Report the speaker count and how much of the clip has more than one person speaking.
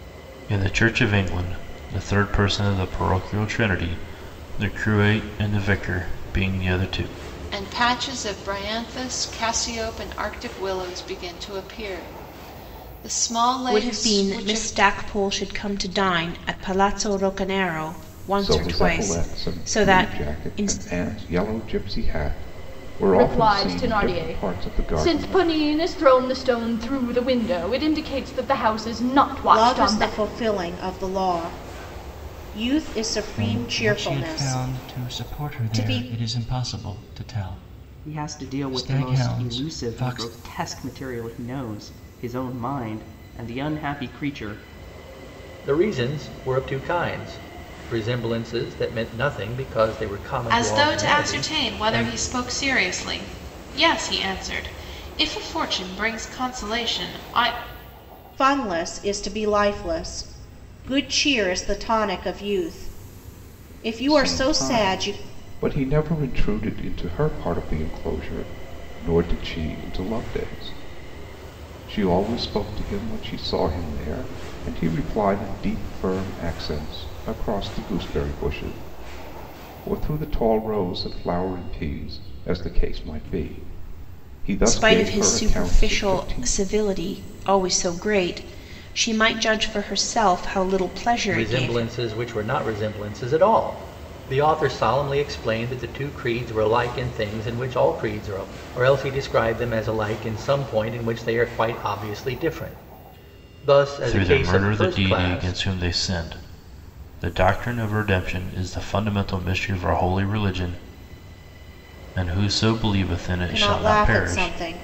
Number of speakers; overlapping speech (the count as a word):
ten, about 17%